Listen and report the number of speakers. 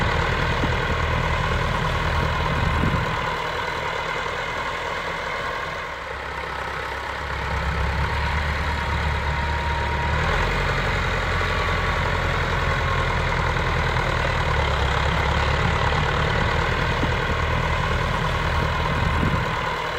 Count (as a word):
zero